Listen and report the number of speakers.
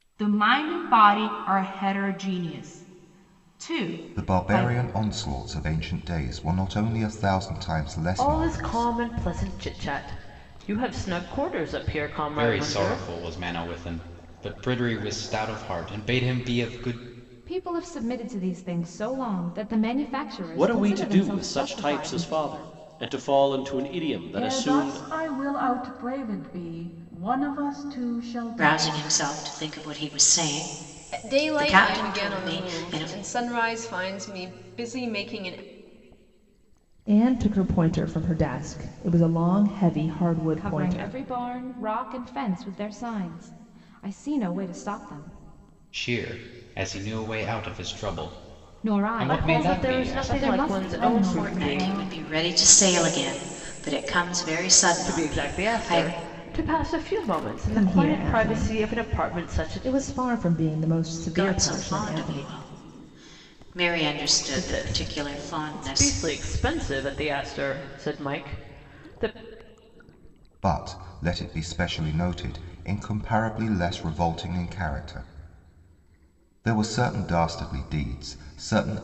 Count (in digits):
10